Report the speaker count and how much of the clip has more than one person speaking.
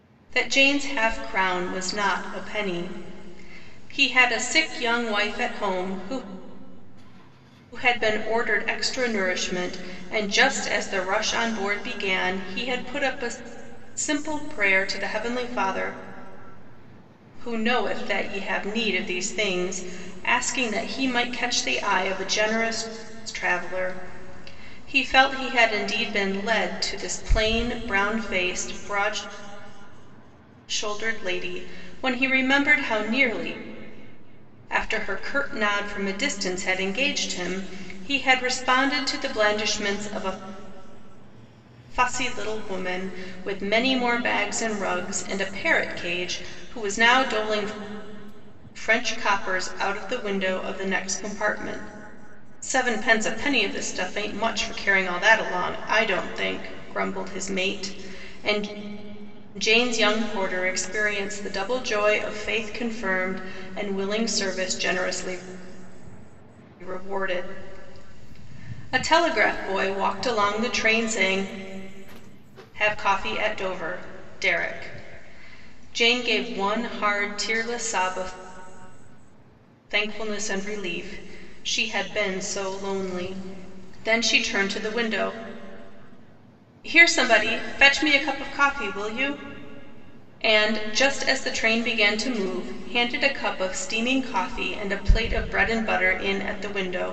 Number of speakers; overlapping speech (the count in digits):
1, no overlap